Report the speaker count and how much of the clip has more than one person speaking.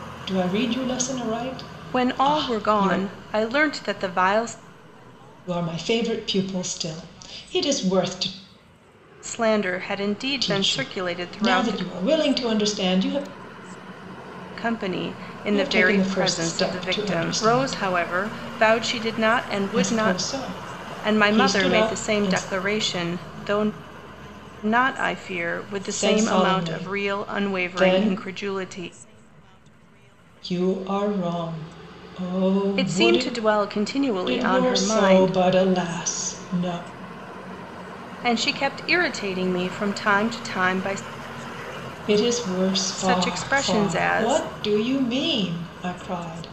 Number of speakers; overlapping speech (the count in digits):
2, about 26%